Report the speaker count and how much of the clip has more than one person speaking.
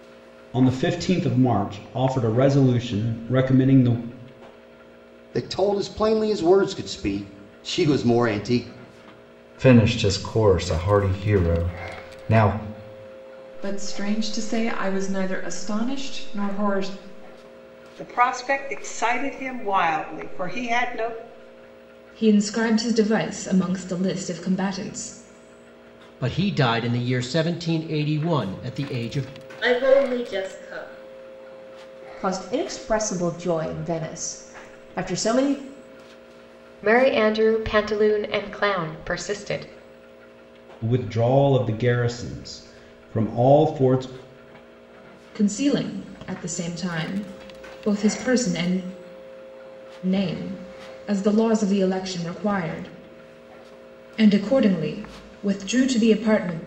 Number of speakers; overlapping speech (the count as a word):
ten, no overlap